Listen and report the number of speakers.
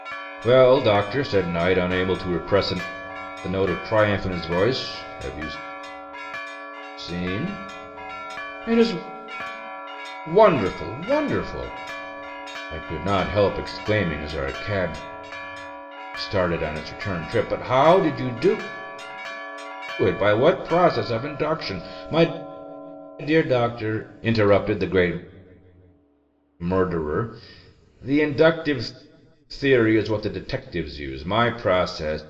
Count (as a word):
one